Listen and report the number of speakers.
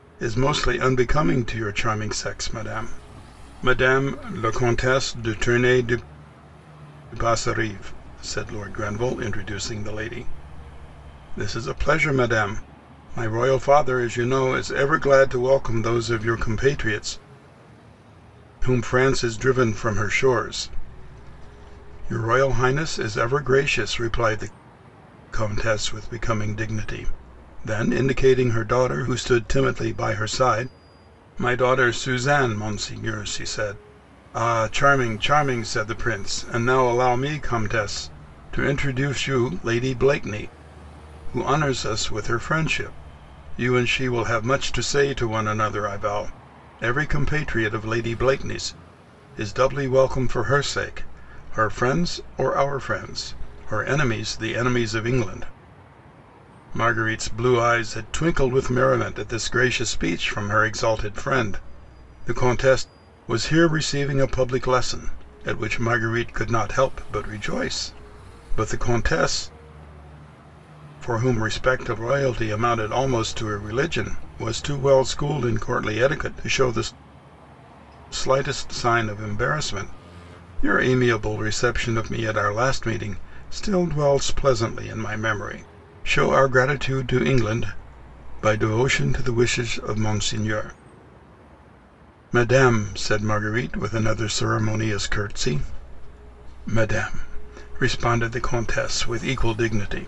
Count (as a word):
one